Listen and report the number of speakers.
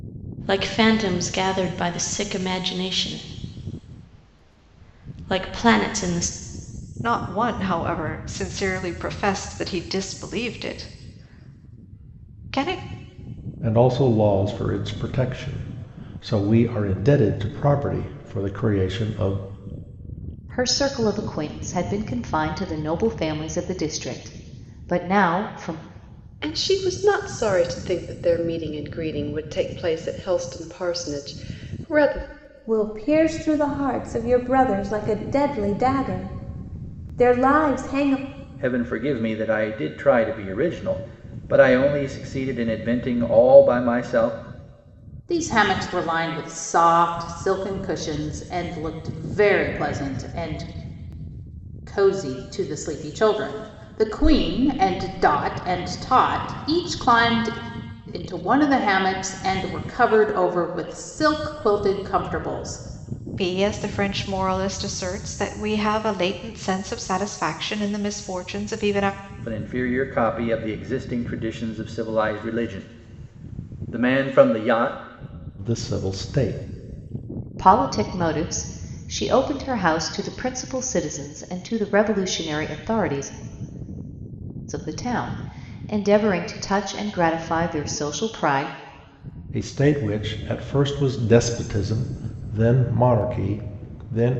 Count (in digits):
8